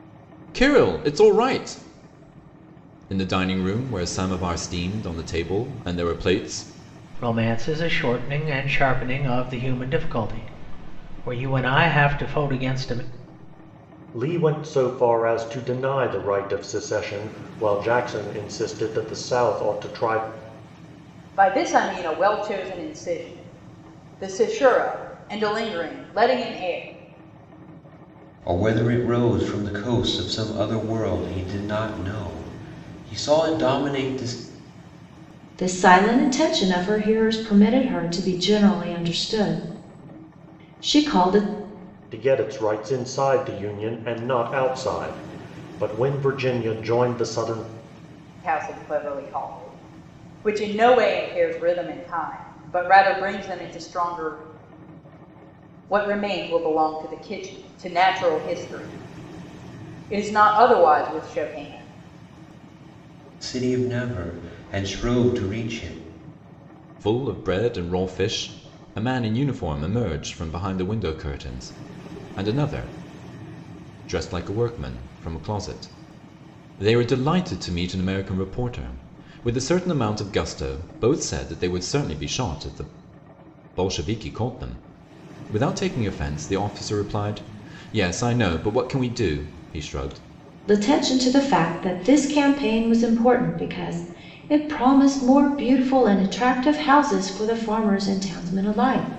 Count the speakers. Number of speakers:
six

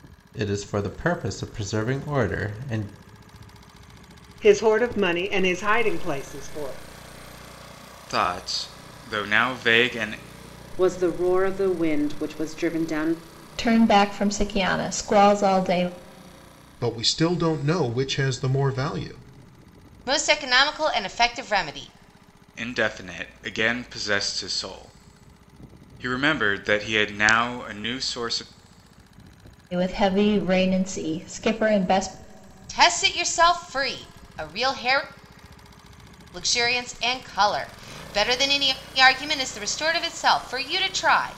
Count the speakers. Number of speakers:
seven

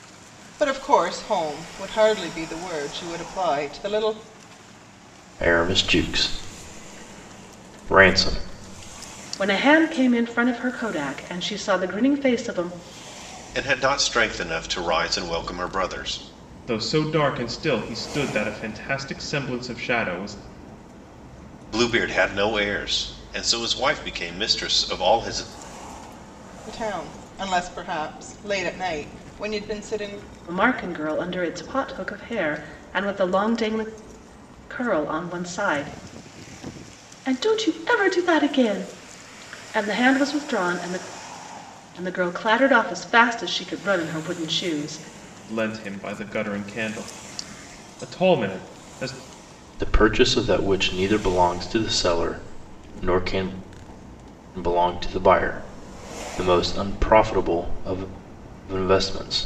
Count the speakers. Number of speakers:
five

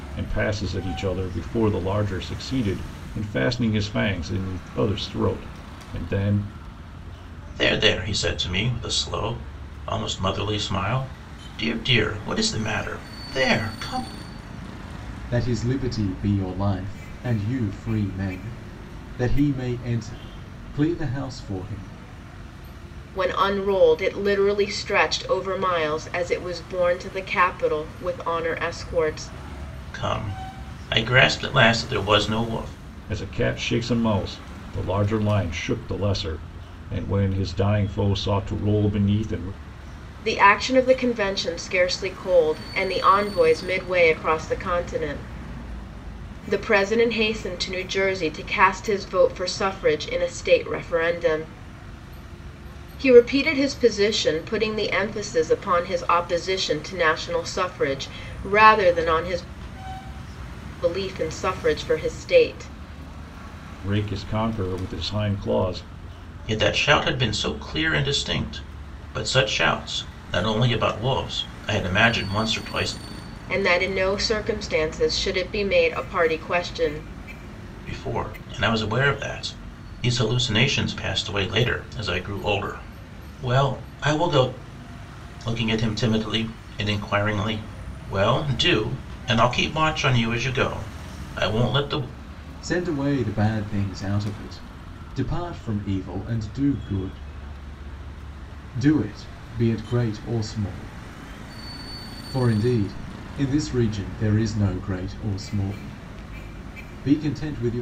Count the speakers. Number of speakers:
four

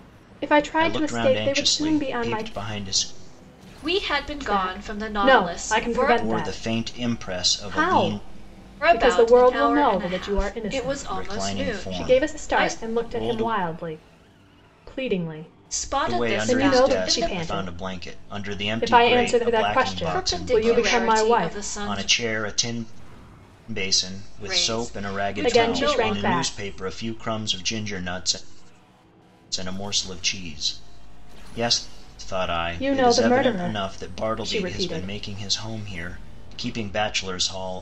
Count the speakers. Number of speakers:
three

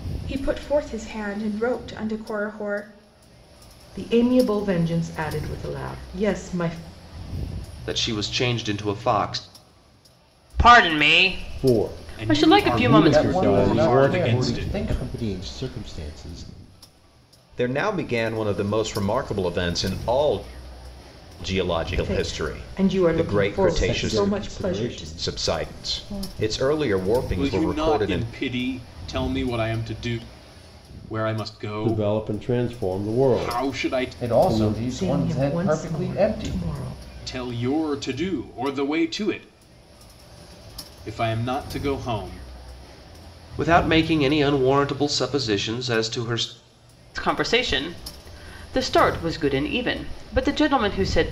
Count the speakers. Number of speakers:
nine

